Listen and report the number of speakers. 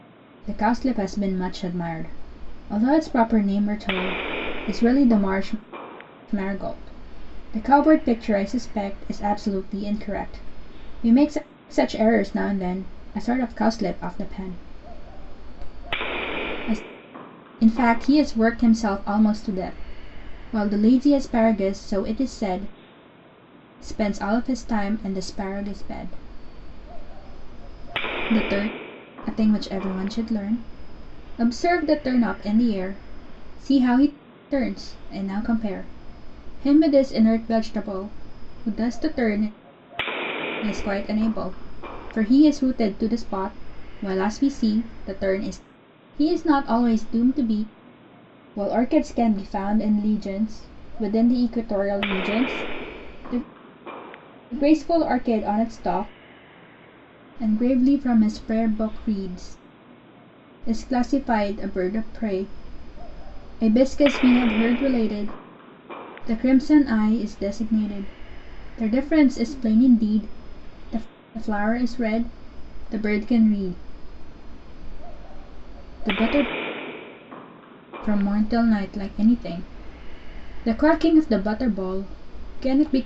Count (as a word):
one